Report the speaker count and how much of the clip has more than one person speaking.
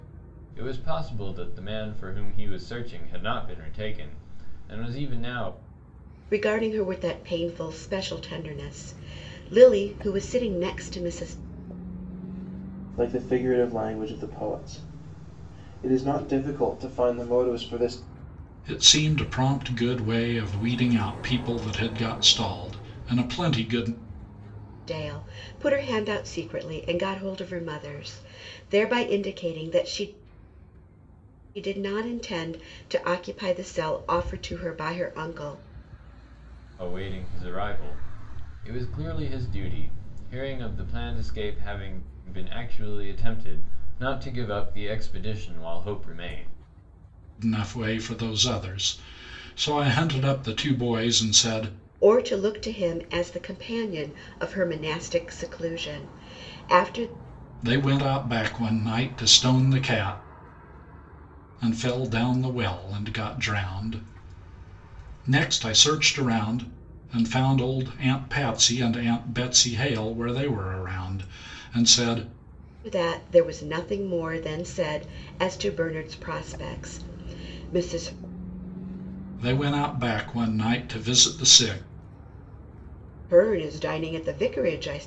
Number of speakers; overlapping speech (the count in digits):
4, no overlap